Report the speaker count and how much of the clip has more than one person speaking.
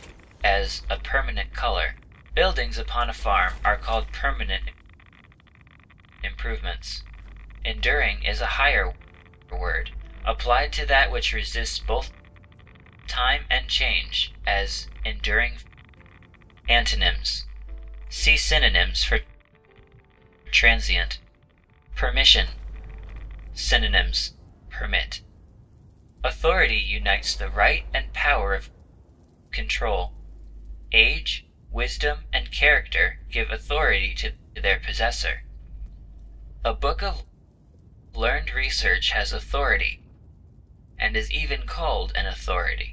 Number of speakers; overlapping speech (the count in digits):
1, no overlap